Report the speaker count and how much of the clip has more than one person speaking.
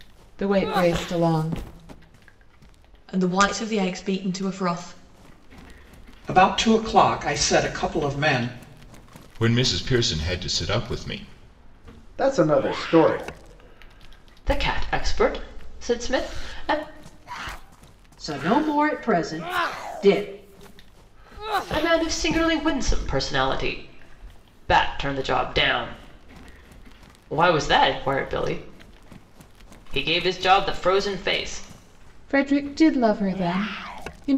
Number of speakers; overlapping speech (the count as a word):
seven, no overlap